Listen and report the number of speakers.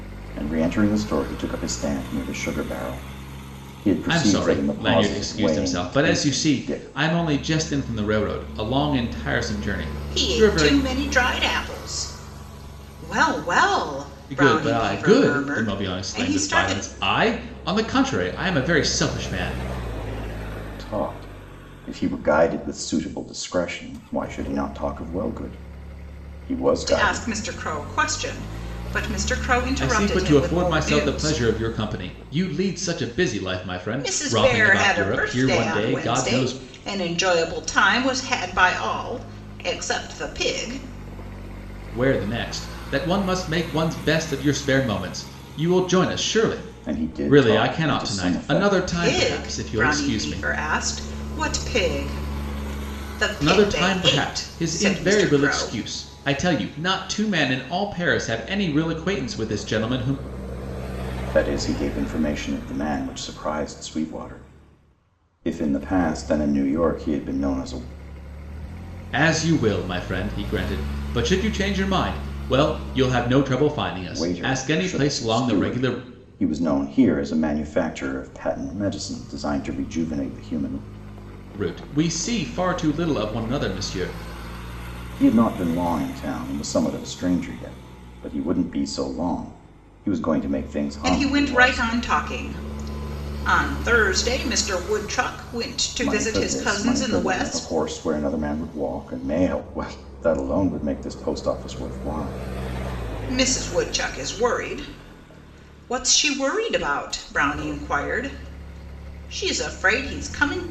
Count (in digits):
3